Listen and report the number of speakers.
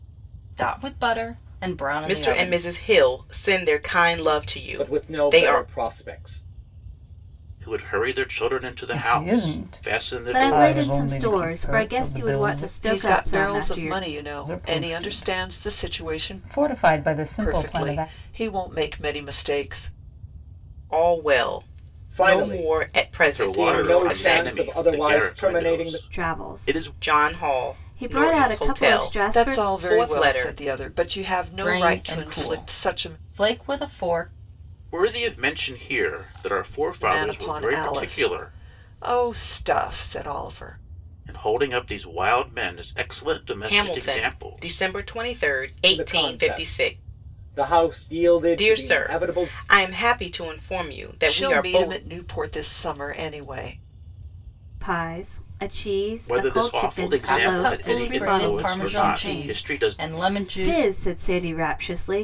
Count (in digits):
7